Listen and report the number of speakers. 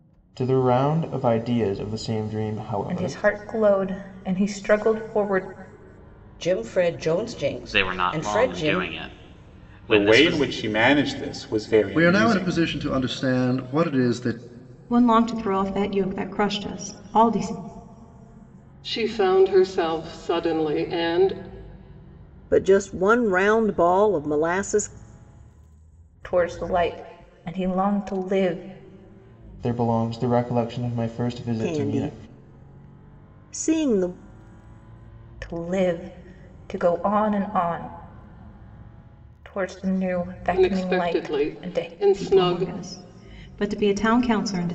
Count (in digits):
9